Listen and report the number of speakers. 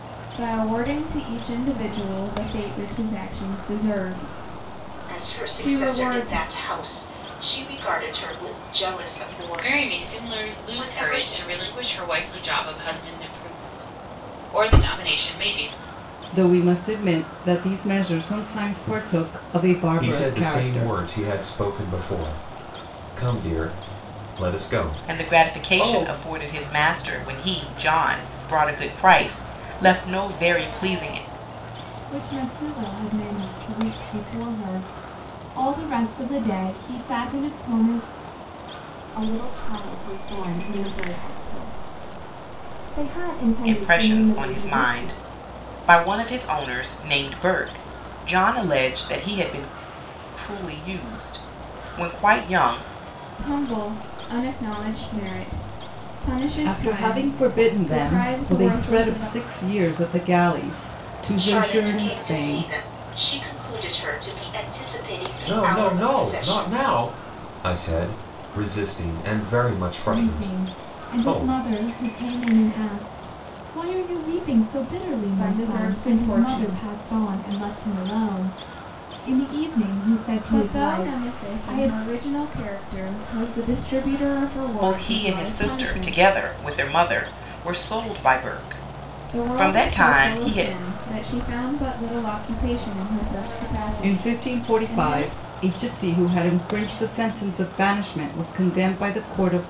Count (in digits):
8